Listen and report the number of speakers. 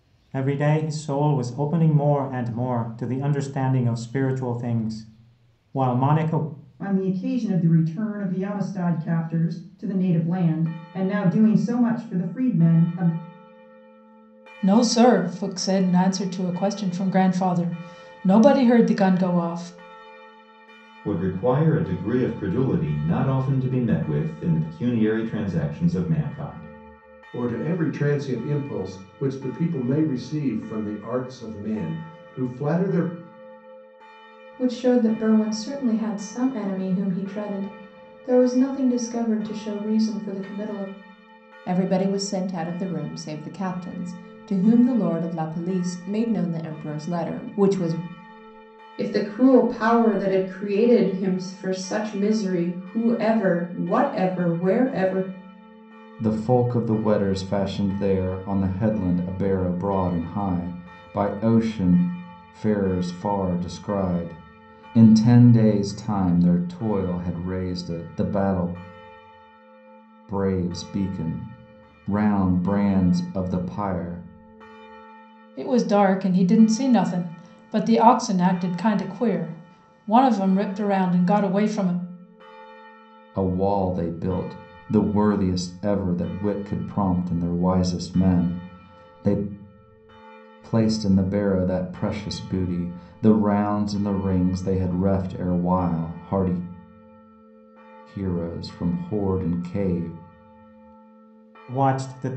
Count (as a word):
nine